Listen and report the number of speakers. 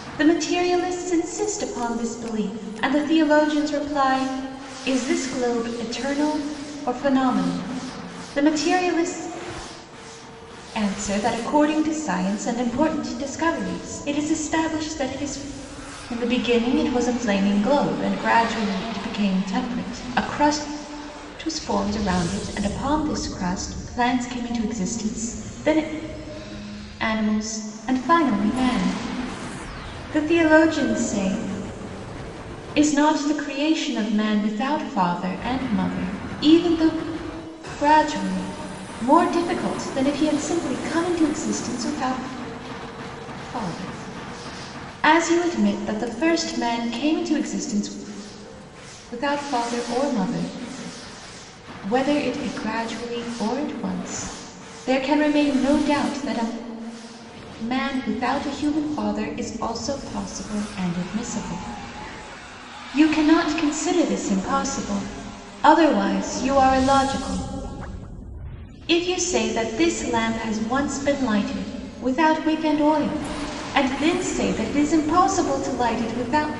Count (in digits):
1